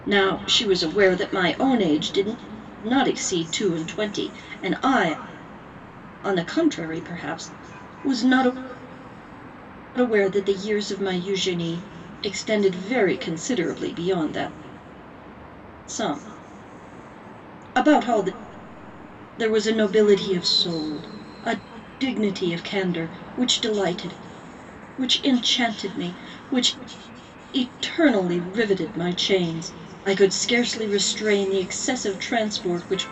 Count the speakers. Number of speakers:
one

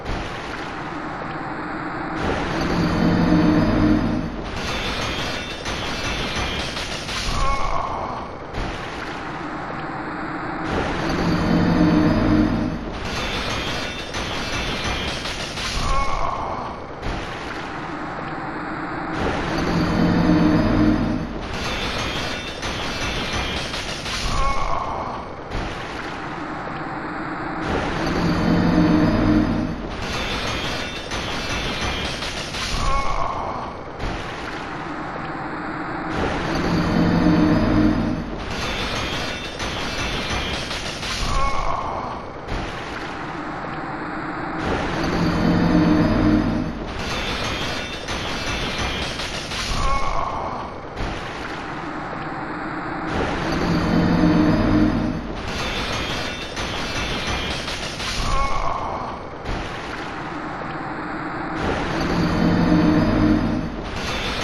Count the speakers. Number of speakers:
zero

